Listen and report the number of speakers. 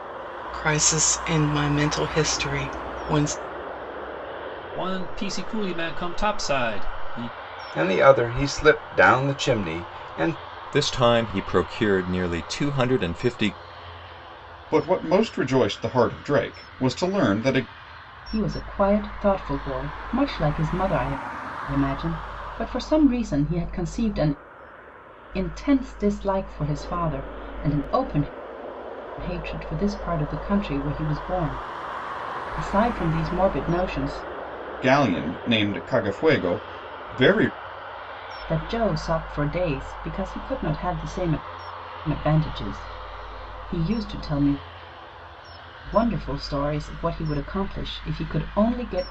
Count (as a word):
six